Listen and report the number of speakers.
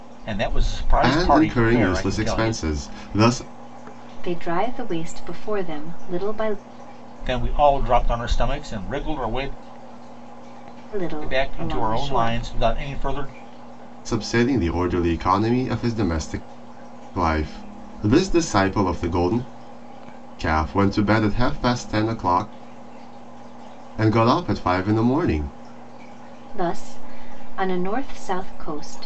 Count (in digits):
3